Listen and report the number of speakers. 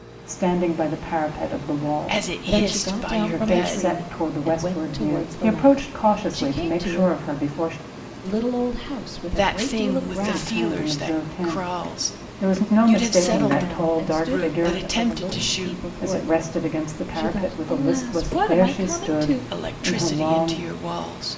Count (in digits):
3